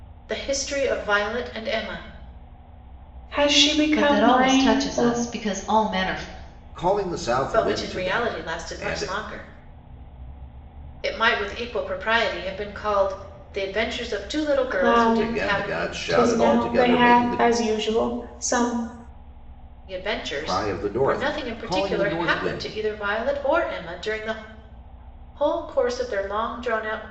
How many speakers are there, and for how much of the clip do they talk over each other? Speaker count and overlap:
4, about 30%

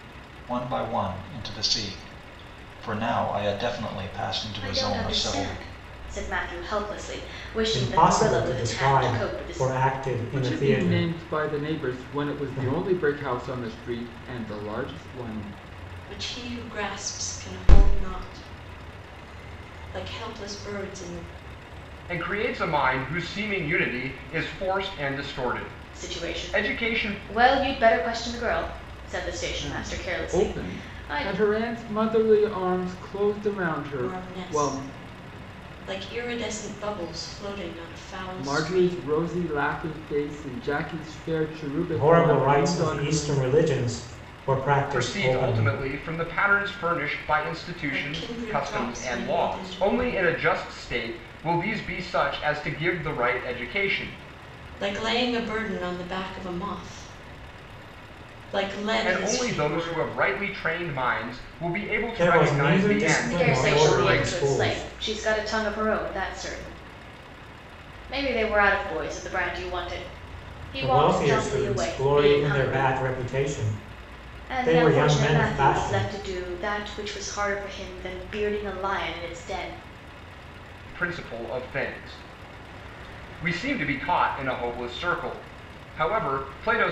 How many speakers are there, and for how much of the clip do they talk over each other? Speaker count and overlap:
6, about 26%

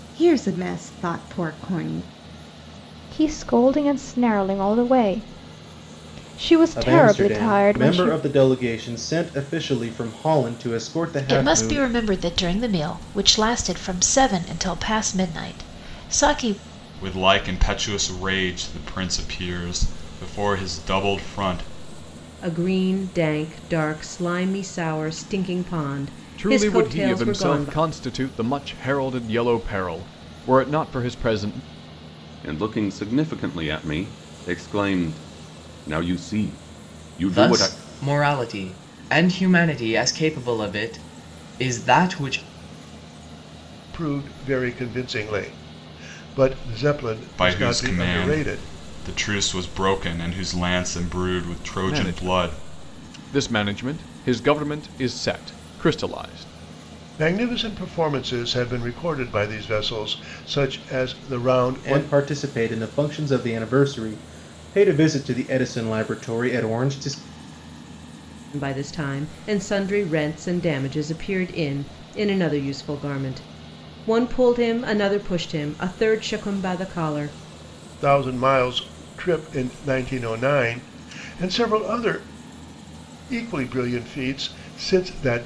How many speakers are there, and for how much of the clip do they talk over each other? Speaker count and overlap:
10, about 7%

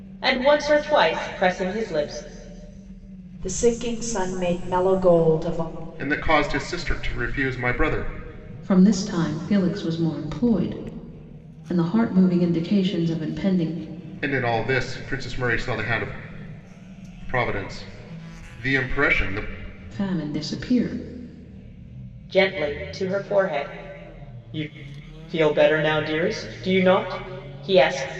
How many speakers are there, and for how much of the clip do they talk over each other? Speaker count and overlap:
4, no overlap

